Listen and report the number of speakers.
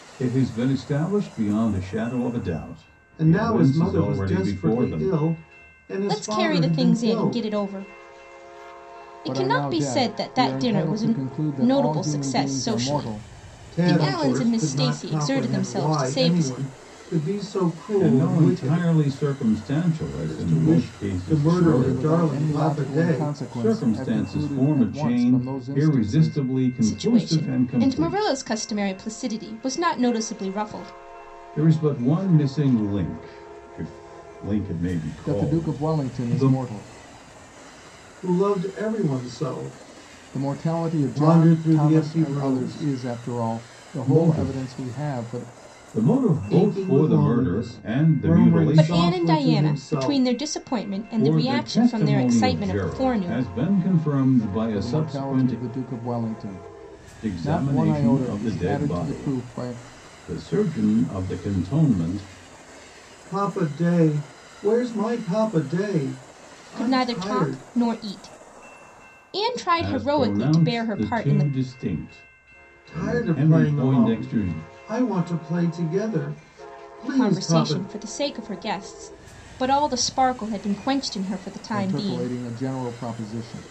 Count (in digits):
4